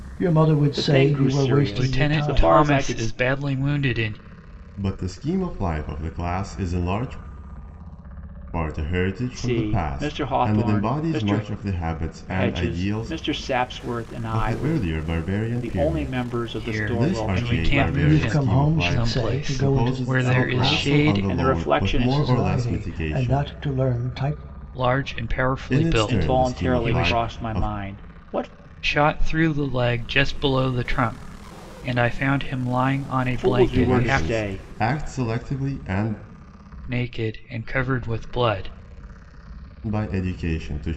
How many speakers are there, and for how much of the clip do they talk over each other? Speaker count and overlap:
4, about 41%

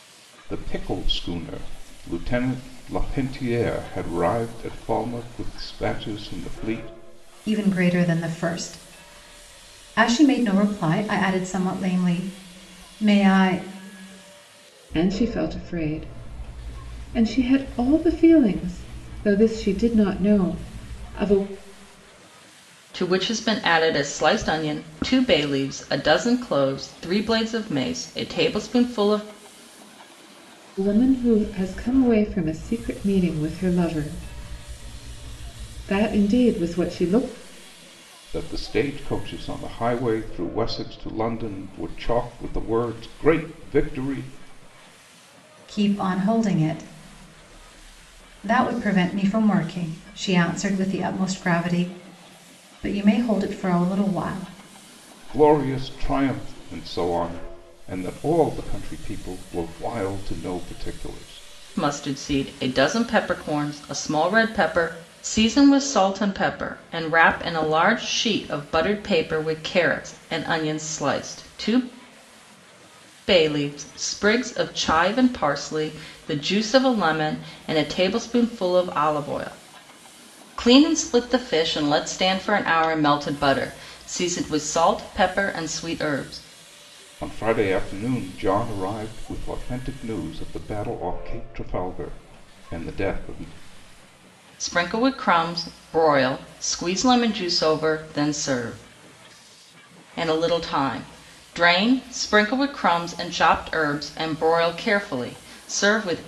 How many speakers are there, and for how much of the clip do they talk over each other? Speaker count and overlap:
4, no overlap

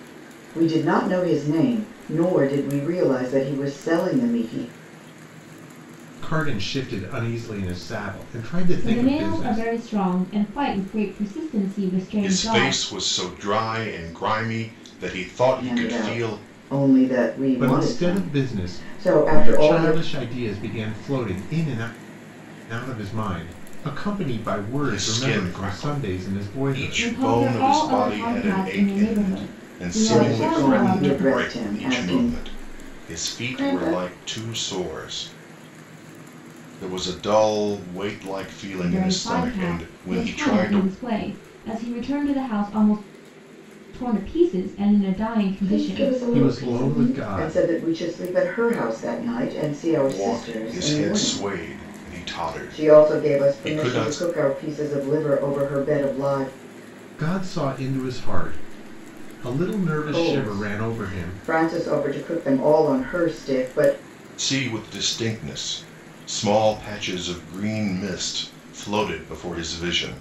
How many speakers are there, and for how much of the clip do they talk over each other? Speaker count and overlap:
4, about 31%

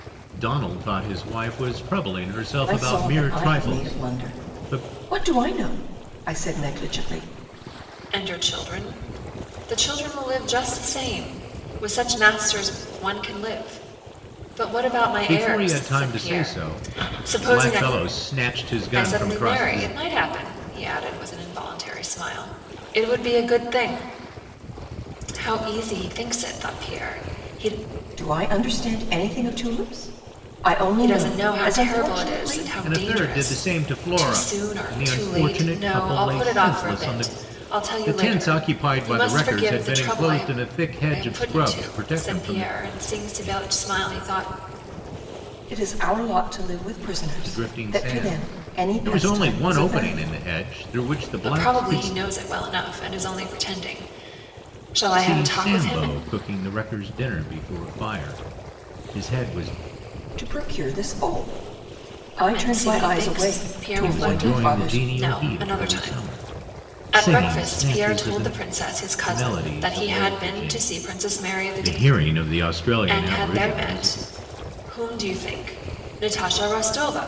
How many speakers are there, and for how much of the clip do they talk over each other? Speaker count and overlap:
3, about 39%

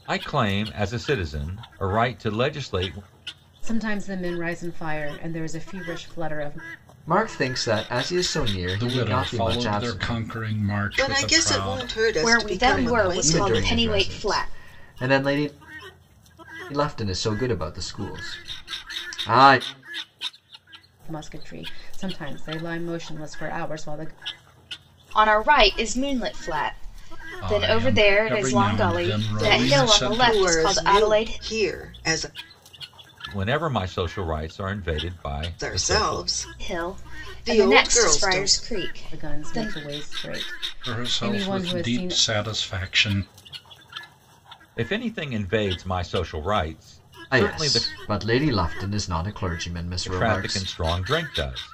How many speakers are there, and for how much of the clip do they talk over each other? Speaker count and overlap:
6, about 29%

